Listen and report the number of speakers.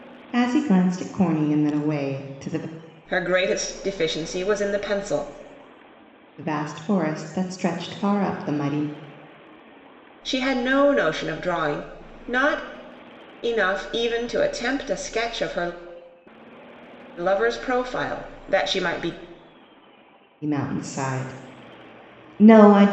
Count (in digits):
2